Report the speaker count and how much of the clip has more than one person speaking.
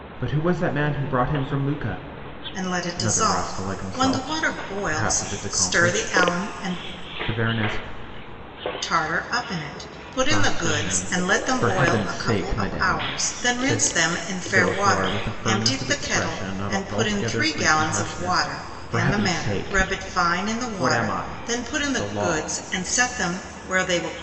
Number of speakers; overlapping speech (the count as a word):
two, about 58%